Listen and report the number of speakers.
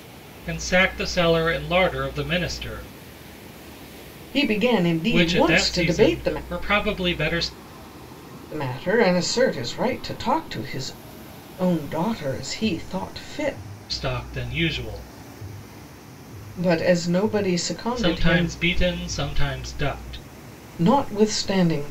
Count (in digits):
2